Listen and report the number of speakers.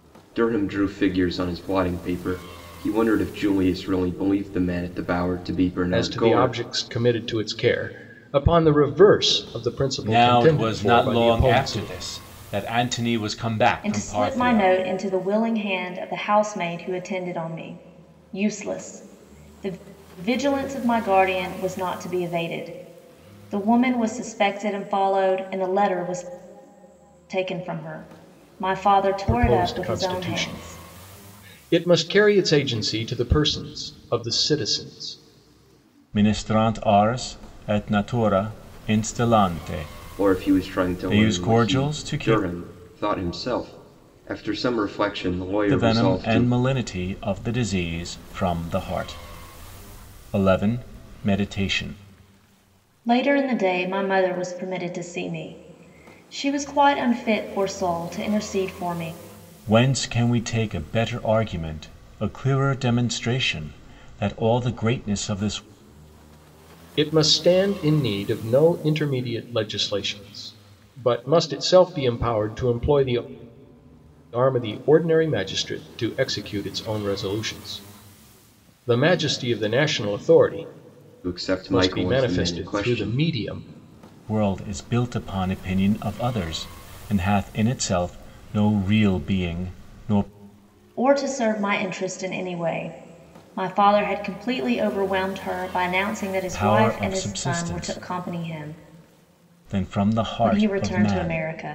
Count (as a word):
four